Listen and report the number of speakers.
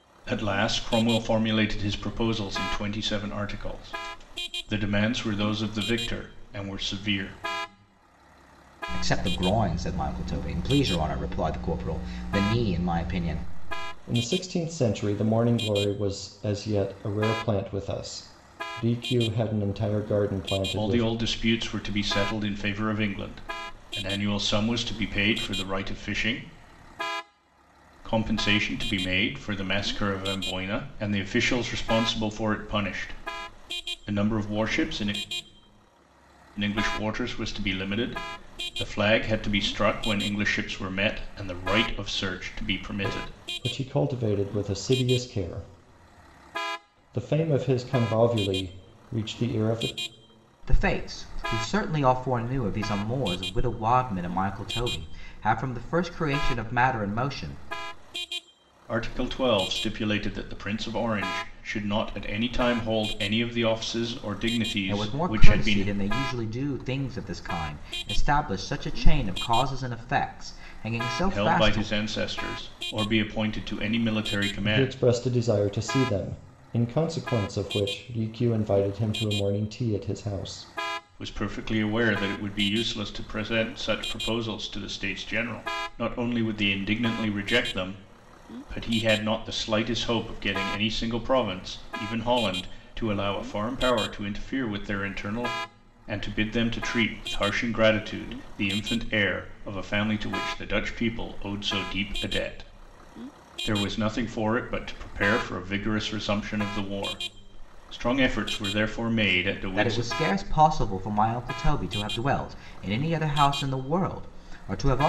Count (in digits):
3